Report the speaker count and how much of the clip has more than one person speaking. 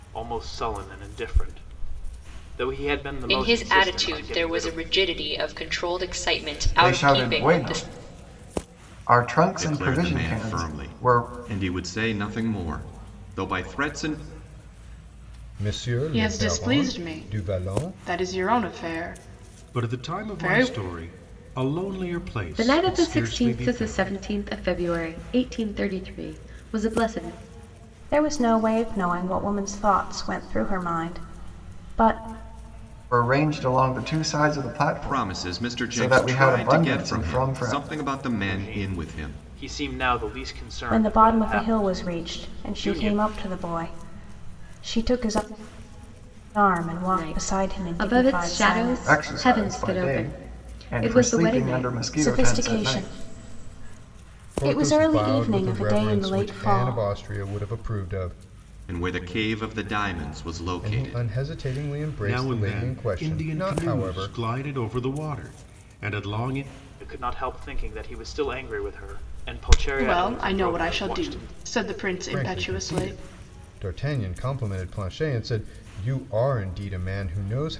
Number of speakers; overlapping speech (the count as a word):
nine, about 37%